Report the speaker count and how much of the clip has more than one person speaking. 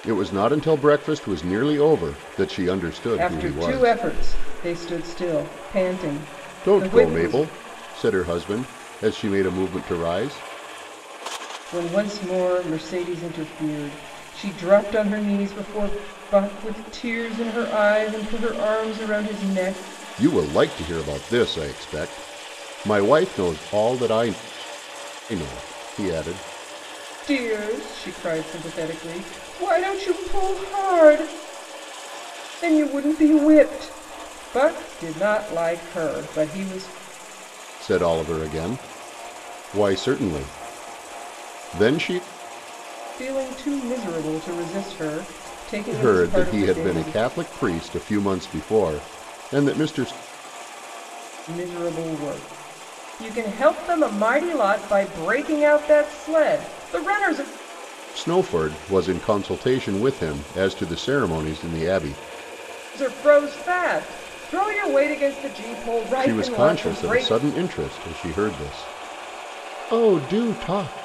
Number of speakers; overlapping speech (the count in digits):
2, about 6%